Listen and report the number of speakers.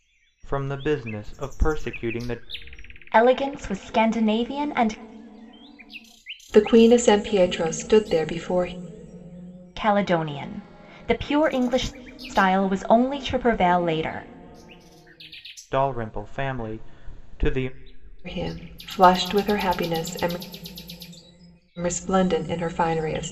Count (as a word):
three